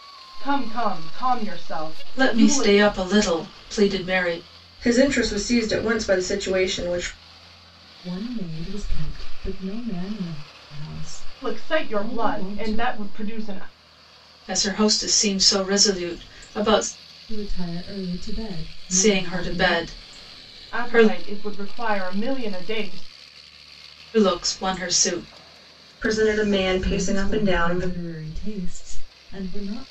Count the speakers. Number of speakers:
4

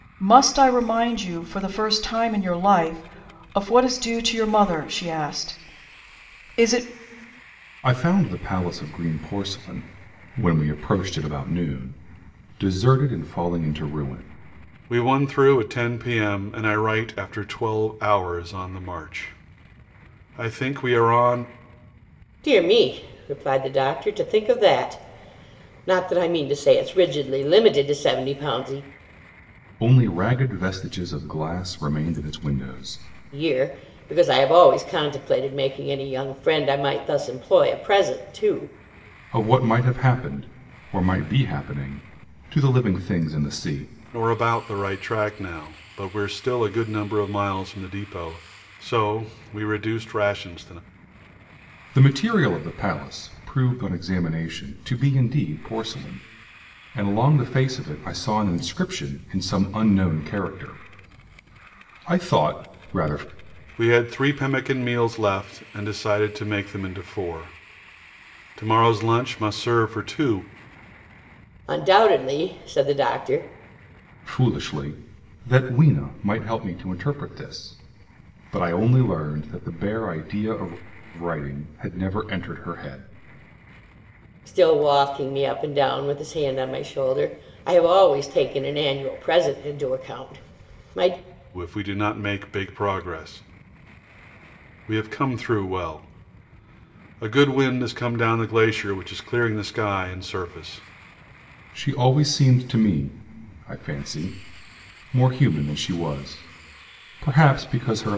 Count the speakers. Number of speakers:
4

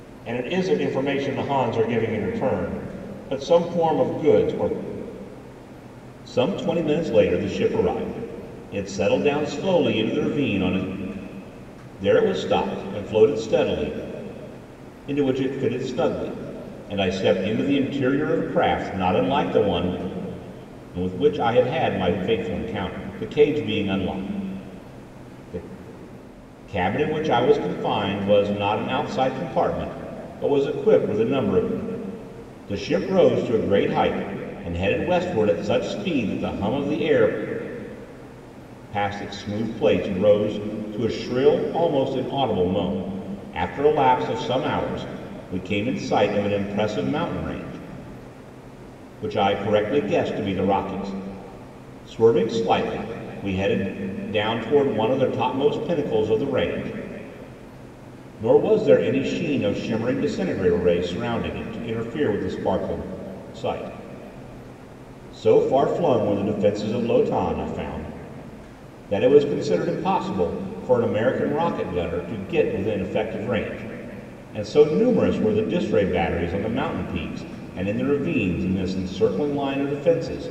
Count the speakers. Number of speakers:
1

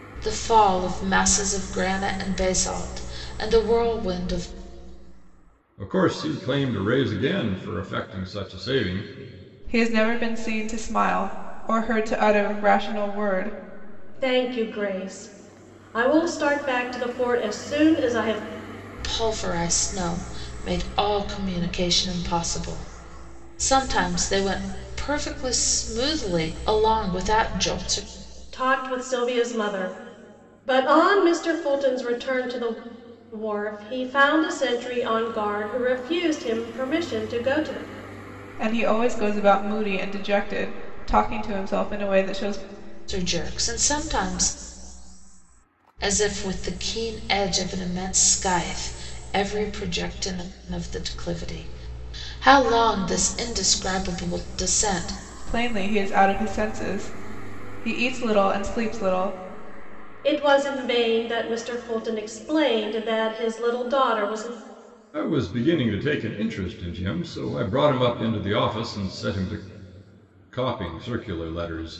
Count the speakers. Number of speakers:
4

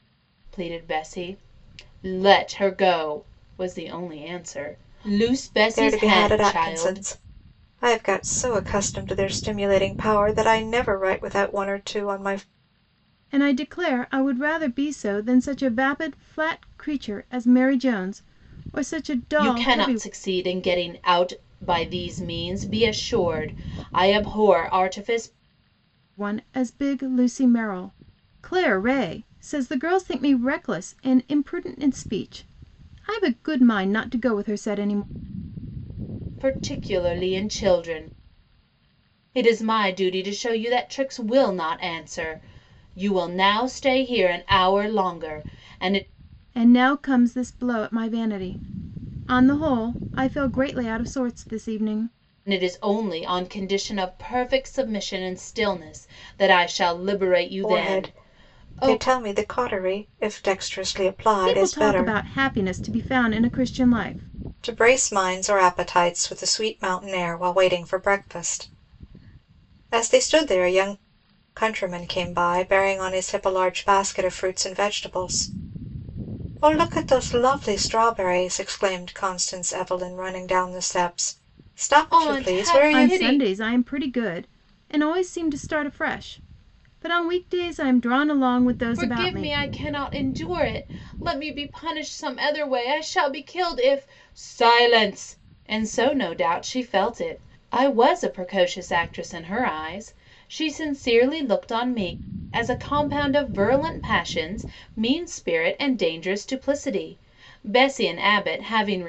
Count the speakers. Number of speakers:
3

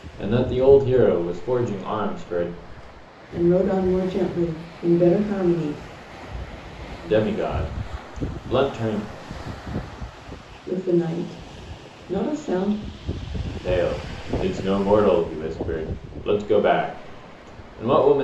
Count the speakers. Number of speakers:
2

